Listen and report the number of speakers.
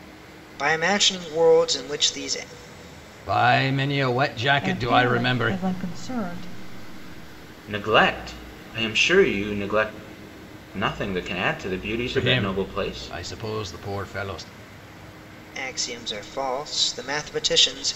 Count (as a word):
four